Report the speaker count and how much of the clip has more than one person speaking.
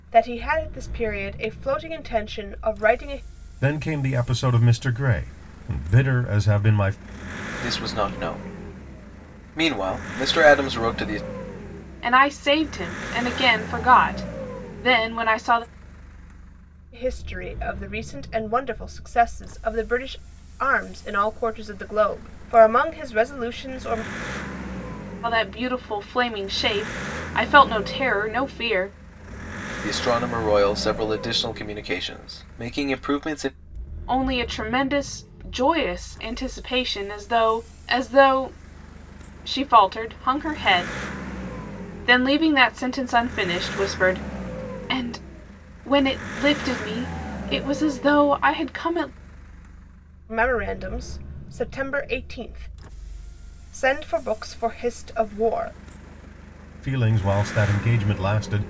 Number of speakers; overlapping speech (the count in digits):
4, no overlap